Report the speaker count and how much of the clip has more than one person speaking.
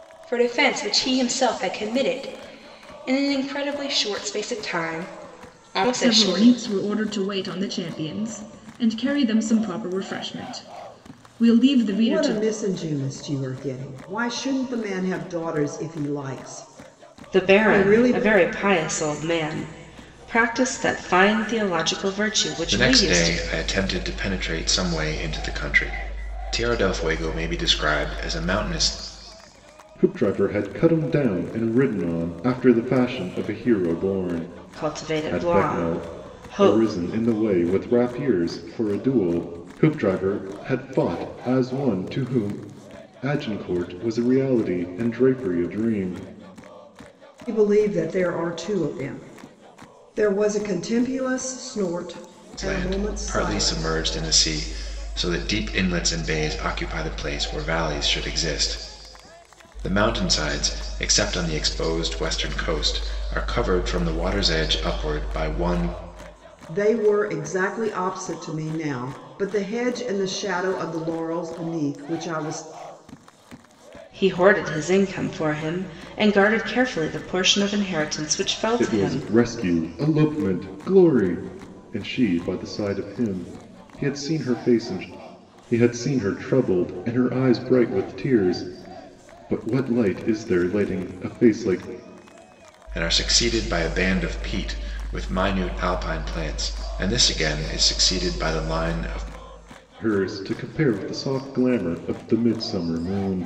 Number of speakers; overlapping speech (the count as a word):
six, about 6%